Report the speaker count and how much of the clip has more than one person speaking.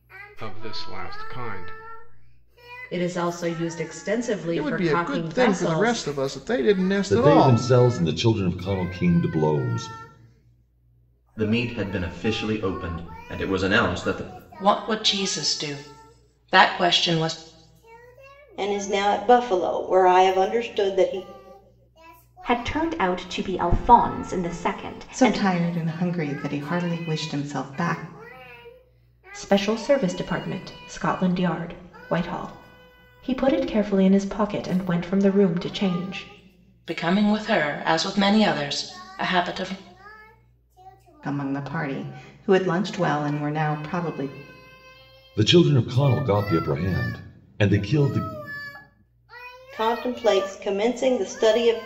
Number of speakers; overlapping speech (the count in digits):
10, about 5%